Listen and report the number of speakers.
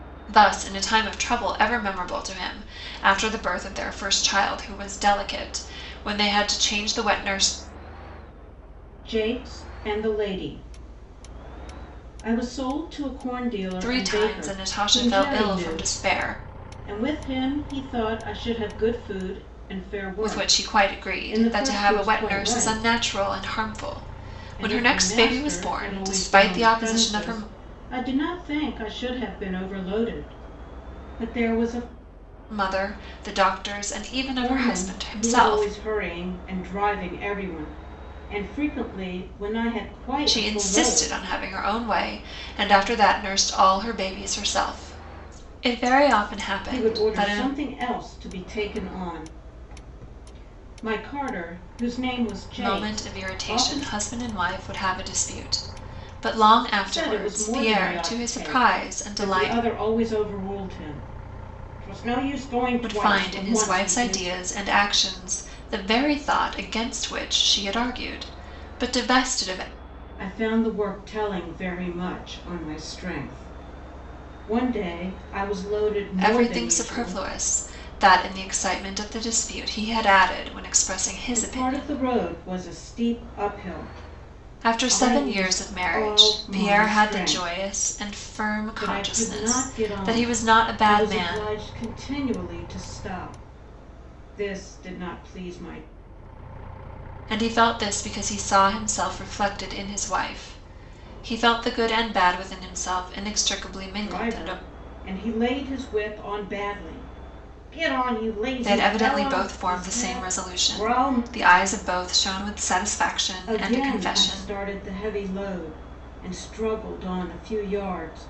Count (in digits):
2